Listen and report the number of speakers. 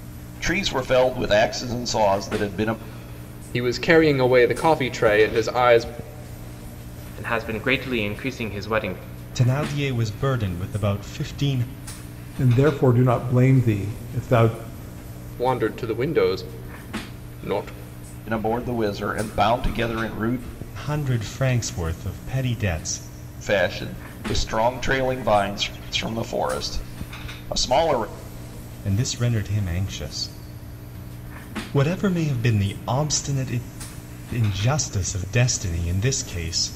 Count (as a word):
five